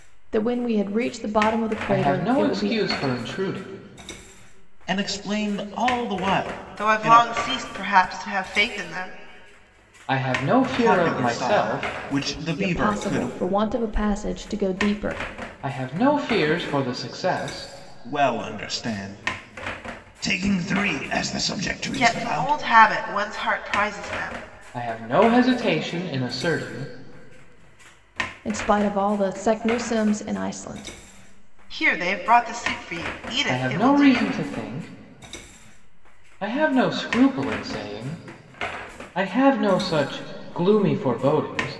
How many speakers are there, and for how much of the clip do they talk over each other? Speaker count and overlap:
four, about 12%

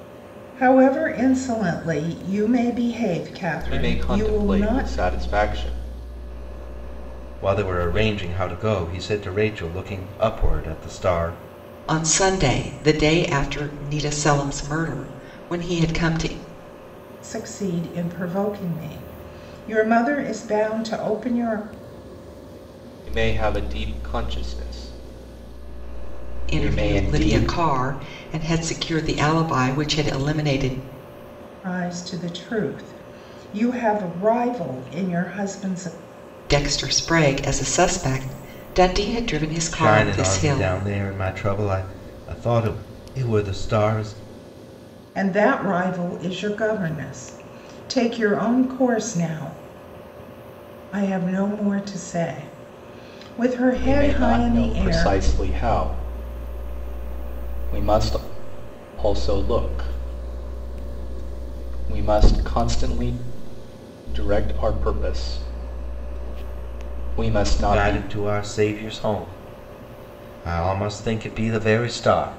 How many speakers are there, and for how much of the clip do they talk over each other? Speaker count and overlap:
four, about 8%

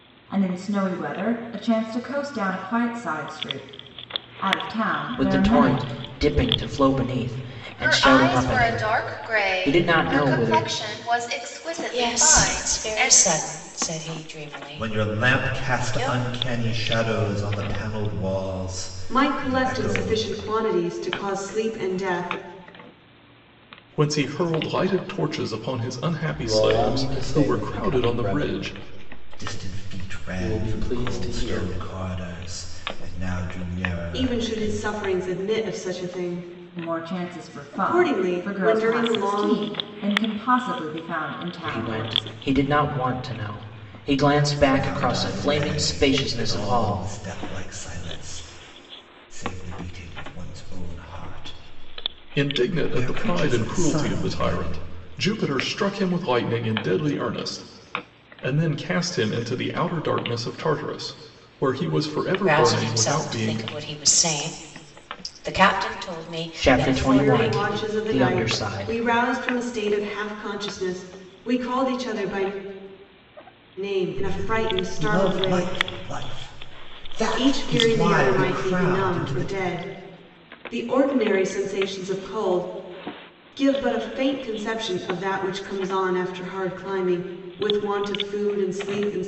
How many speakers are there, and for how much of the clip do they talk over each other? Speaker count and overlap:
eight, about 32%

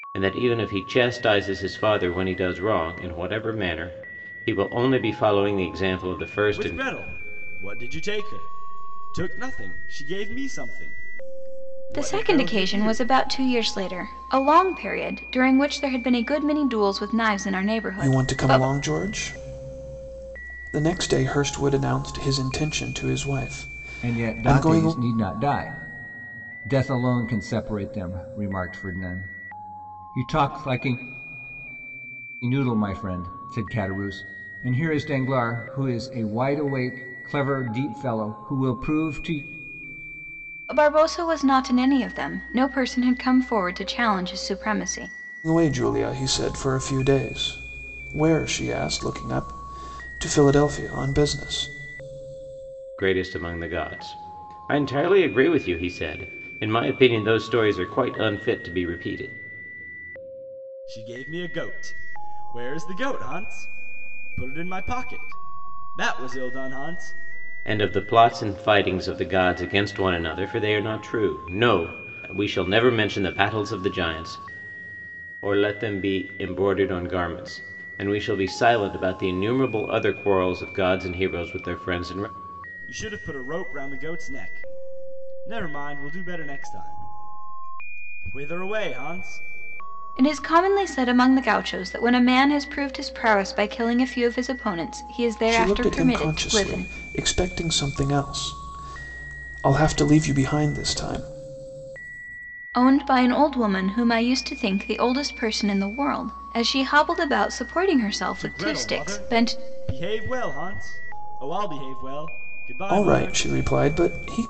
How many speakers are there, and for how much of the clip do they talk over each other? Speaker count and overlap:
five, about 6%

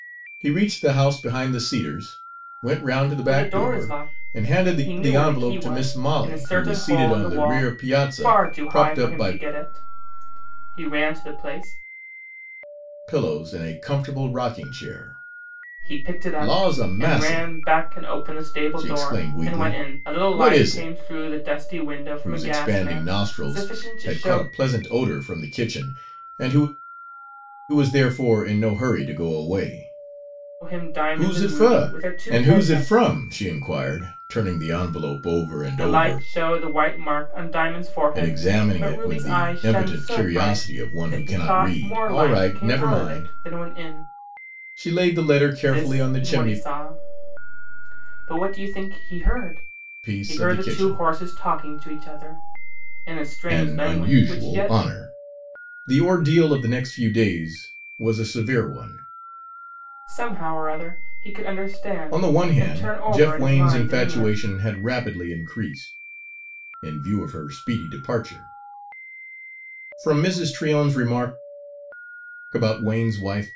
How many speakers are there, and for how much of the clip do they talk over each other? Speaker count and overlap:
two, about 35%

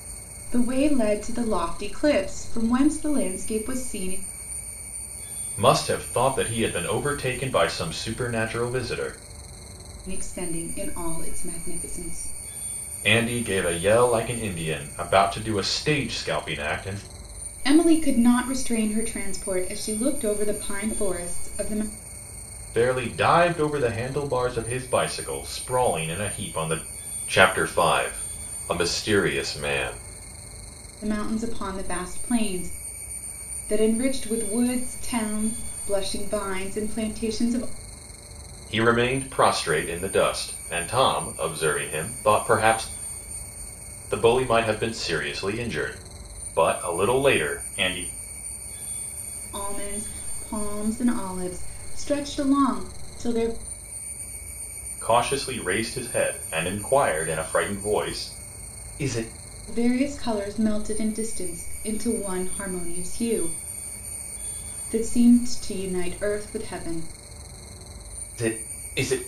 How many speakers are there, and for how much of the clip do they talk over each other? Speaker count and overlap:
two, no overlap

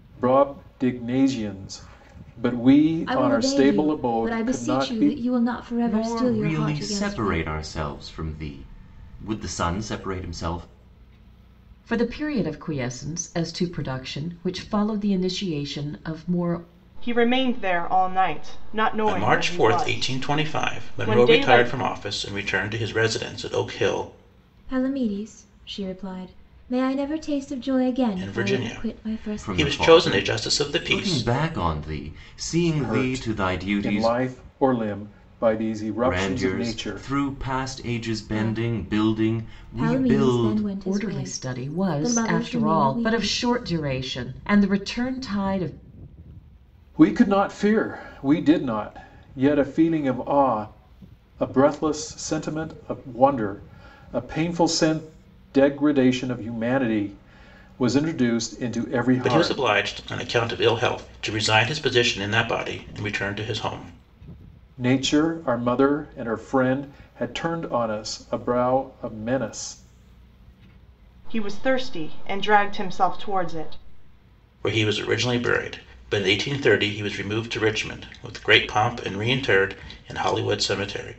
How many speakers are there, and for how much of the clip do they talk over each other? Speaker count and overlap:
six, about 22%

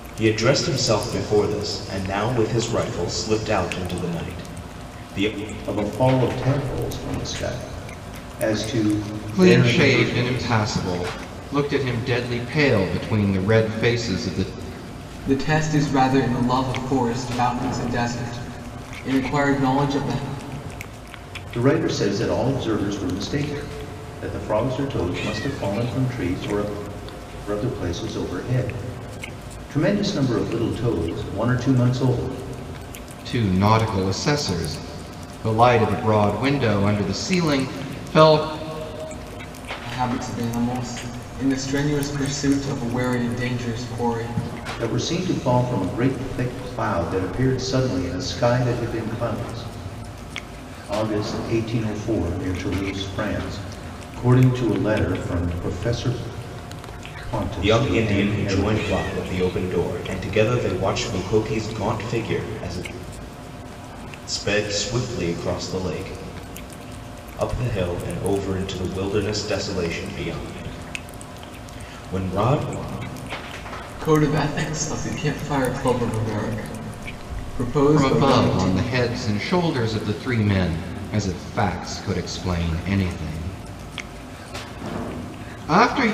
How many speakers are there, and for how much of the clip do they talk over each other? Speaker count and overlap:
four, about 4%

